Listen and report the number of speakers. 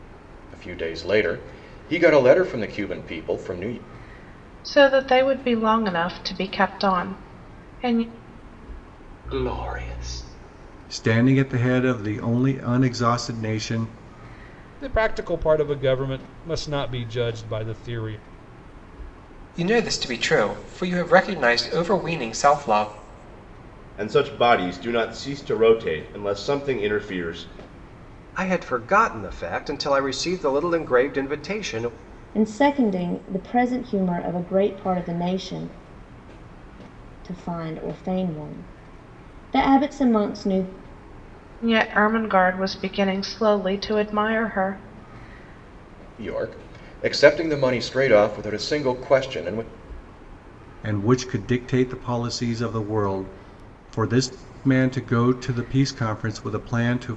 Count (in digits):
9